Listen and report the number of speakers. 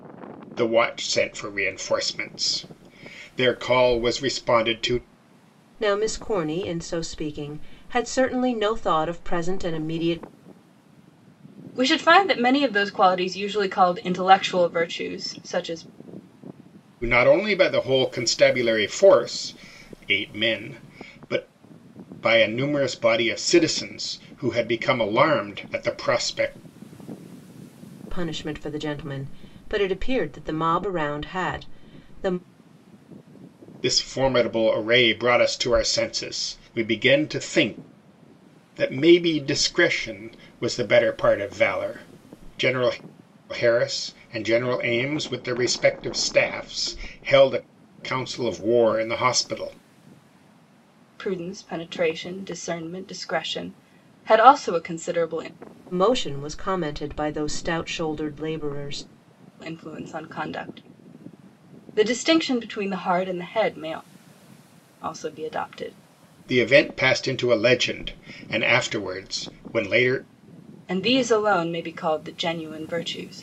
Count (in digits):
3